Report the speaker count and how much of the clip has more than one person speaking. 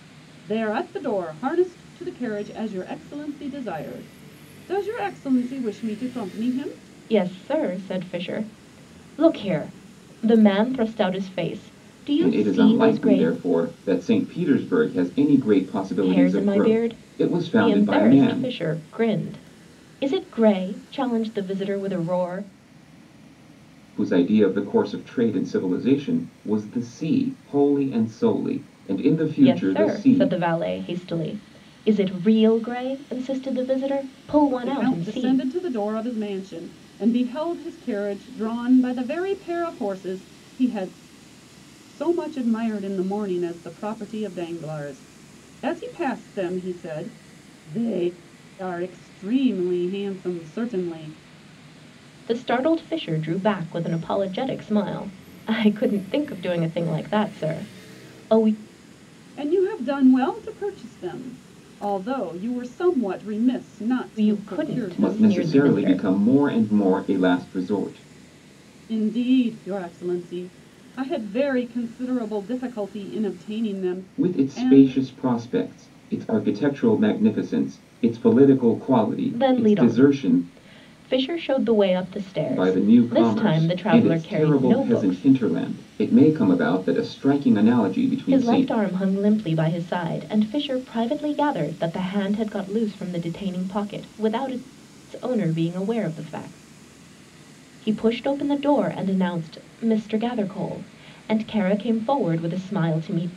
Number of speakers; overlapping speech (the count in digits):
3, about 12%